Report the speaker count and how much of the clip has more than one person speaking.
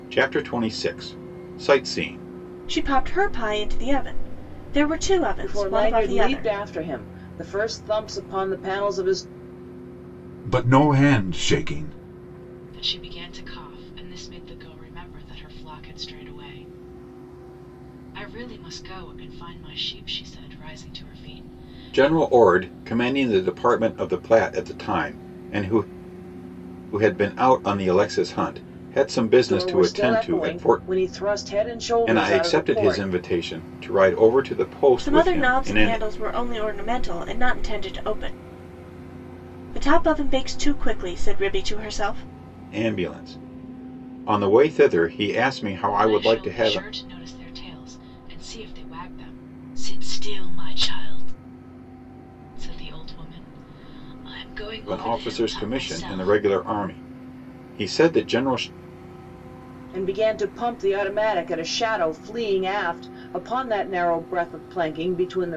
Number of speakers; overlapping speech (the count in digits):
5, about 12%